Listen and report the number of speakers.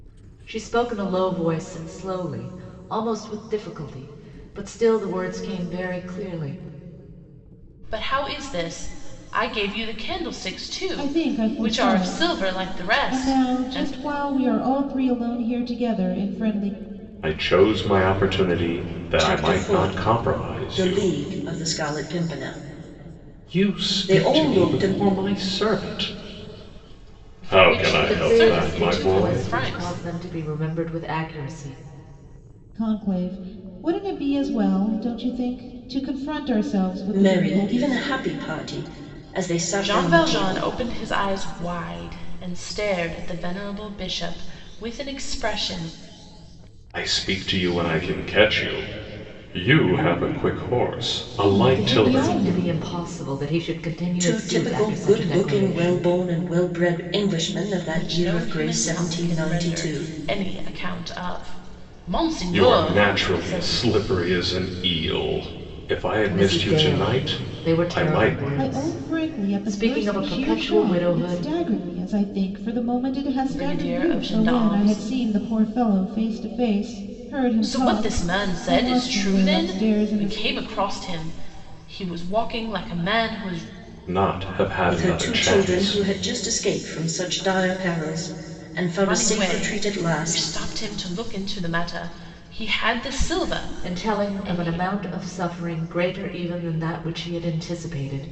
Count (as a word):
five